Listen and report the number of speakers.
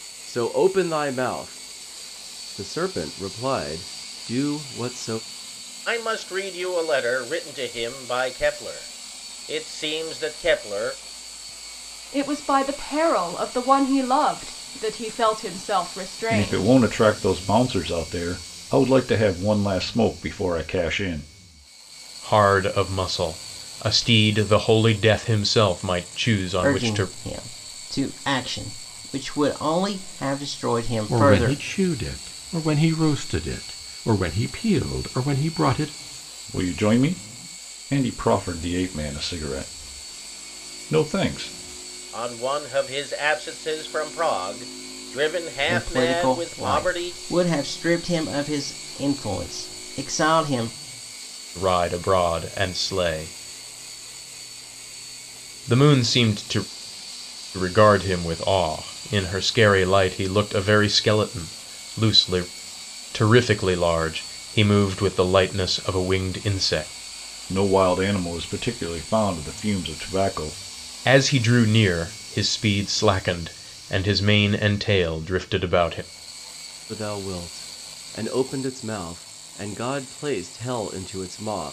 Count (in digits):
7